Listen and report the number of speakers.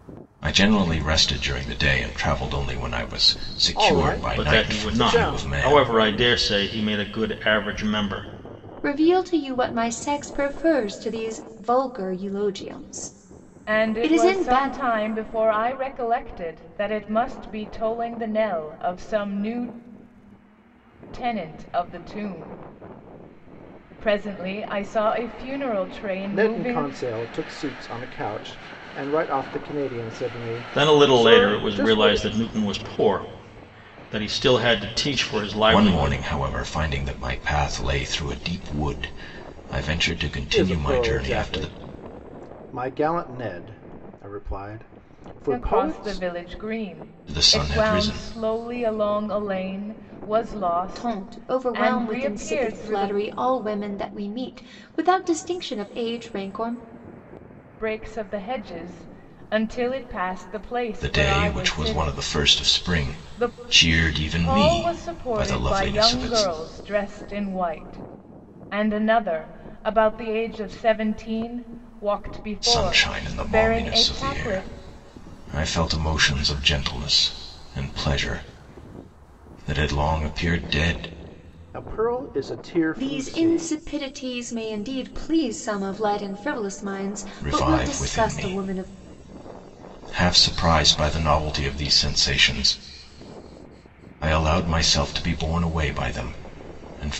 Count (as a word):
five